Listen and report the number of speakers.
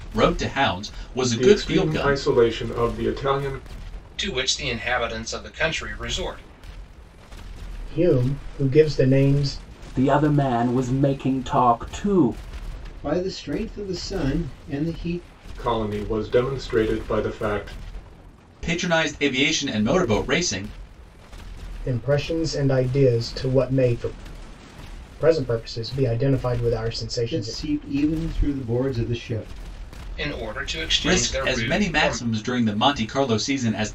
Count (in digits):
6